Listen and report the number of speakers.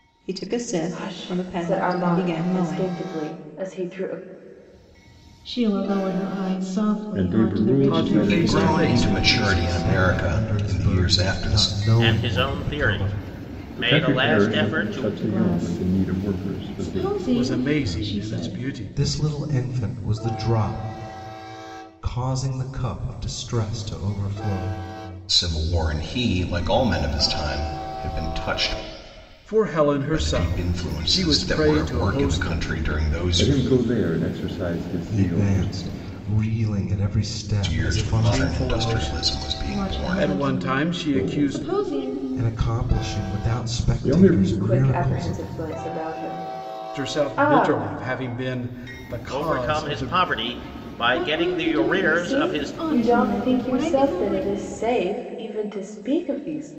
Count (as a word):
eight